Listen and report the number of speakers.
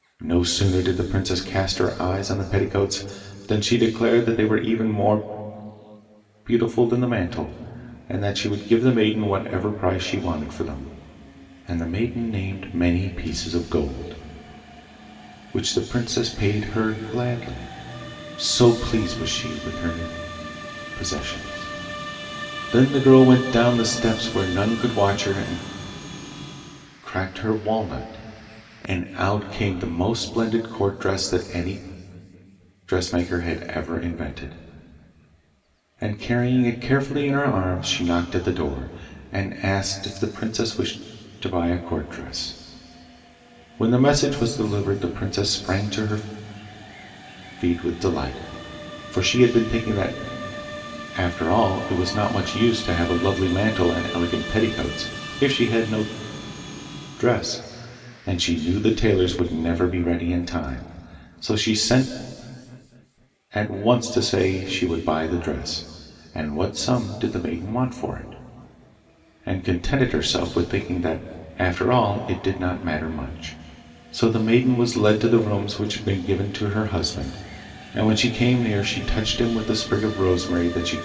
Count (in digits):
1